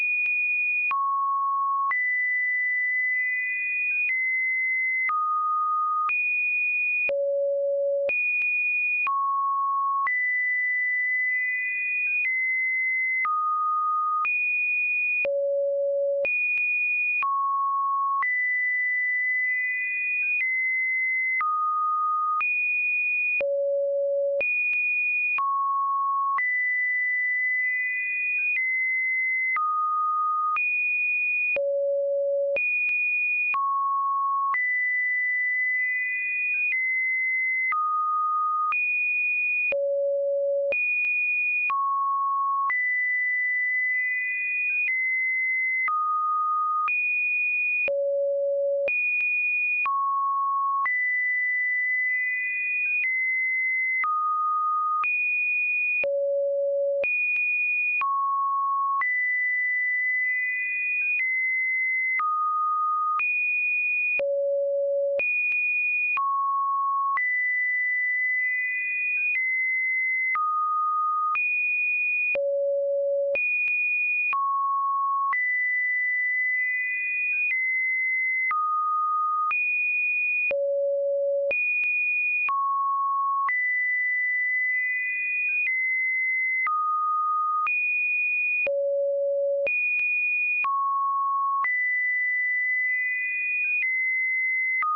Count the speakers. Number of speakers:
0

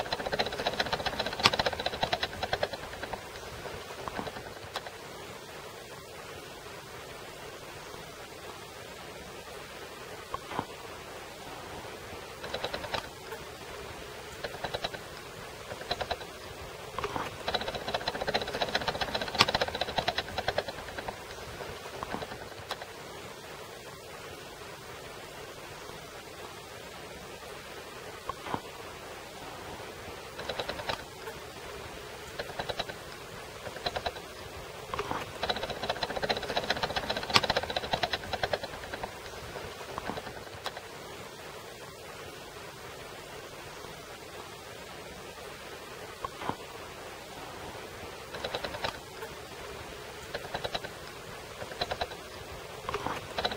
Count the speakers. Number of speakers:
0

